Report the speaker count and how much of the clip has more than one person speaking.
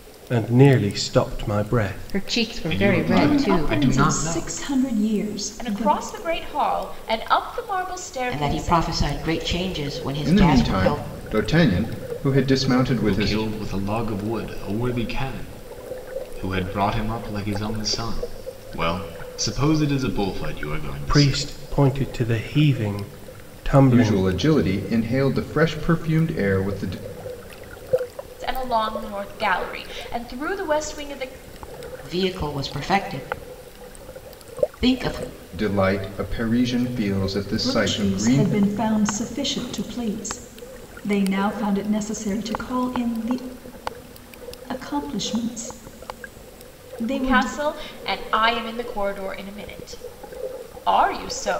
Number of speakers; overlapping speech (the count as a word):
seven, about 13%